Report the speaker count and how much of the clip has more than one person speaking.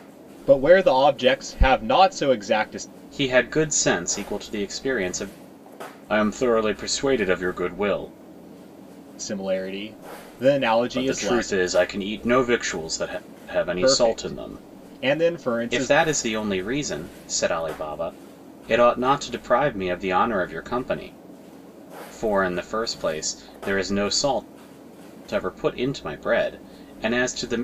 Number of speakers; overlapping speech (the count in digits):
2, about 7%